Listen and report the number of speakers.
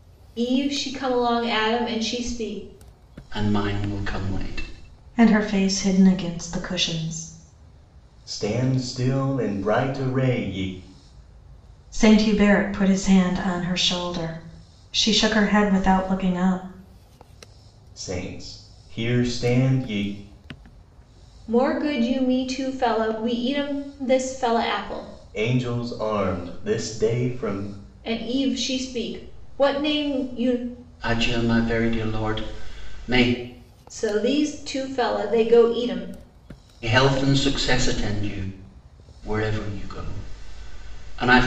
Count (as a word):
four